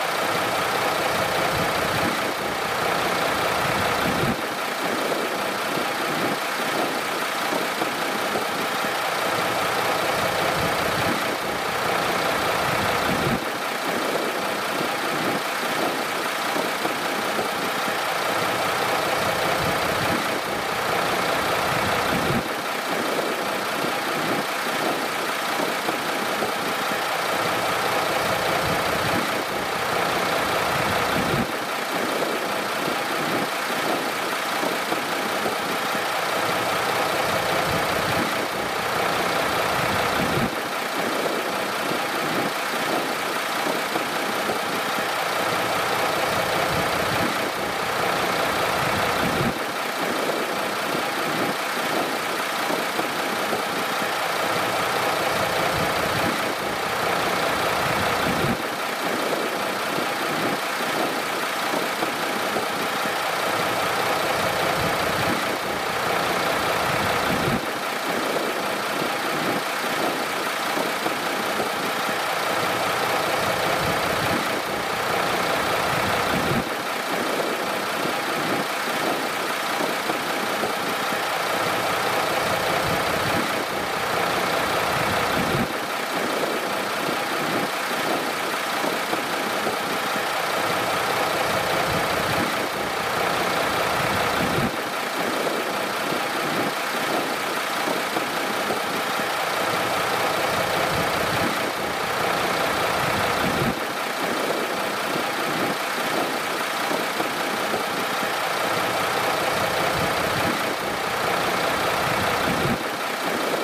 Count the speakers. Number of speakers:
0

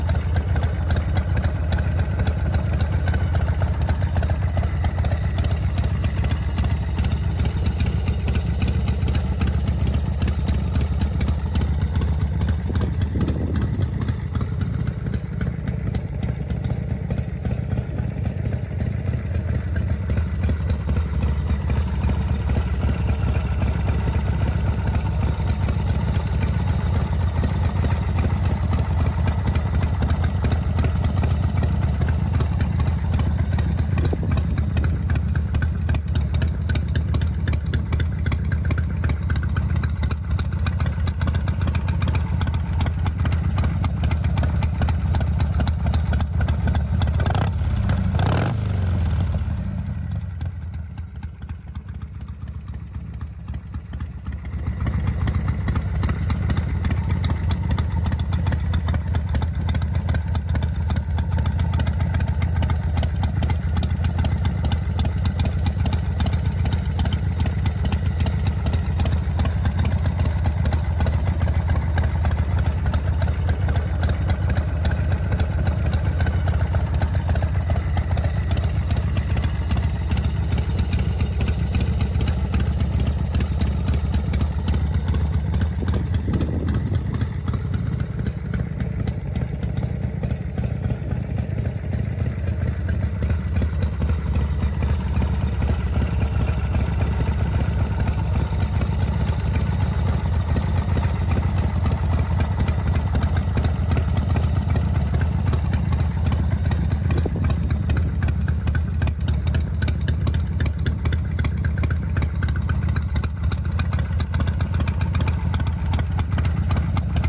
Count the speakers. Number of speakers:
0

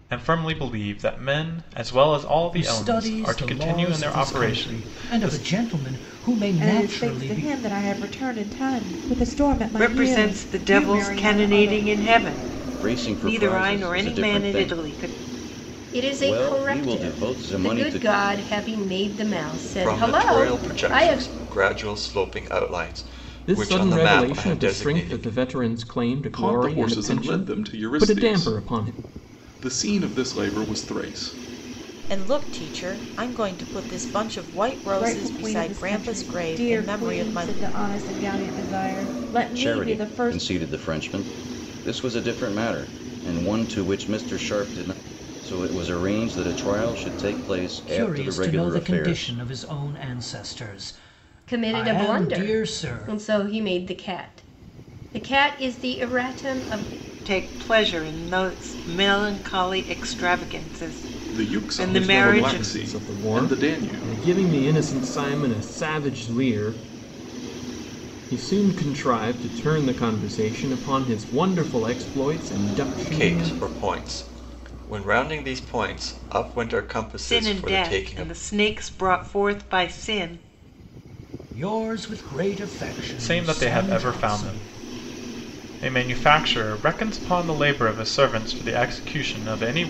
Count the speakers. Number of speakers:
10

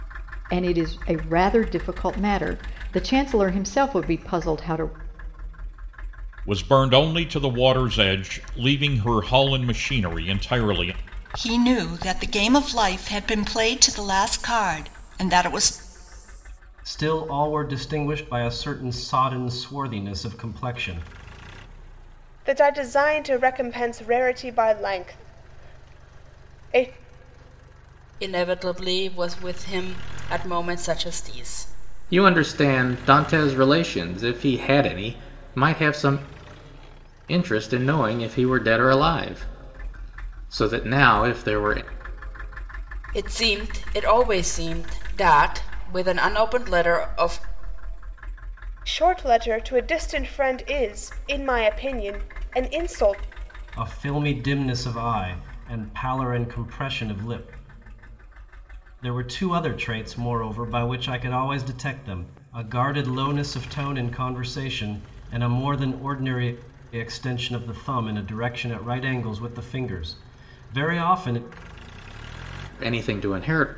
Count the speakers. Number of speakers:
7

